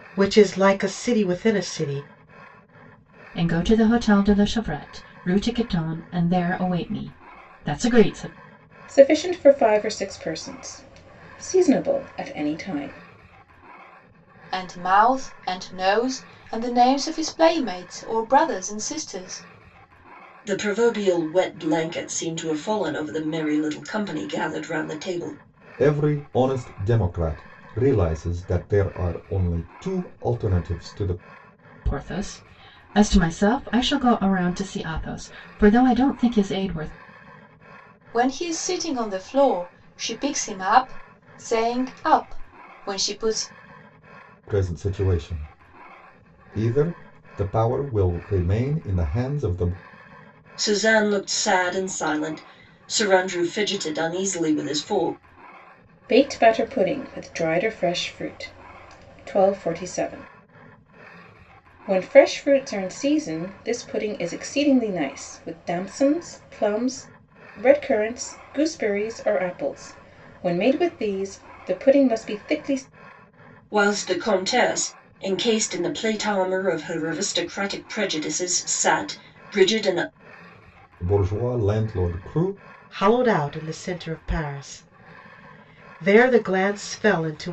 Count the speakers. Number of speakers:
6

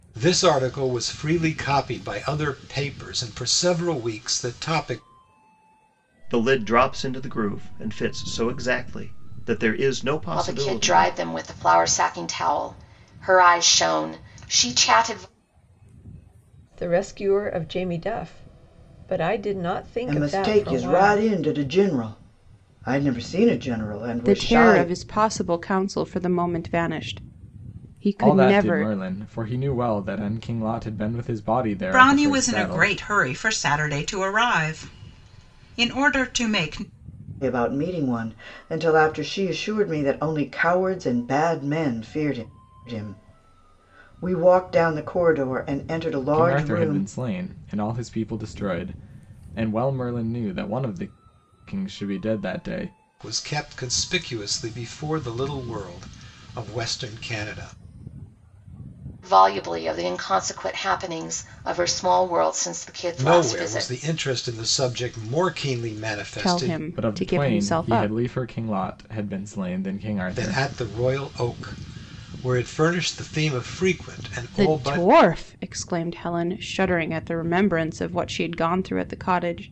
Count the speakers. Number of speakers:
8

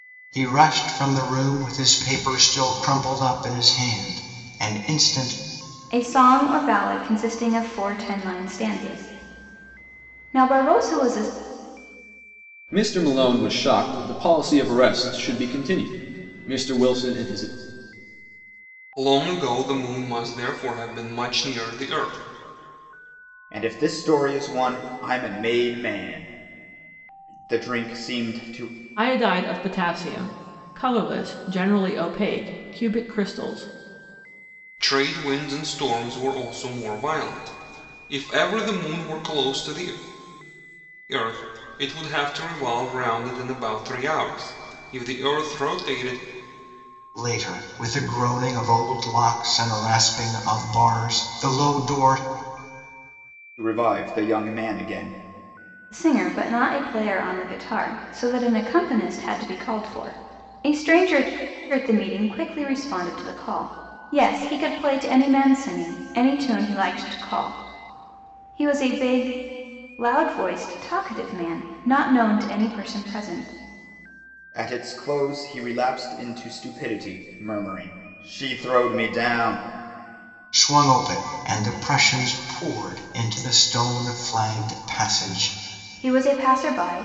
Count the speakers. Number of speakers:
6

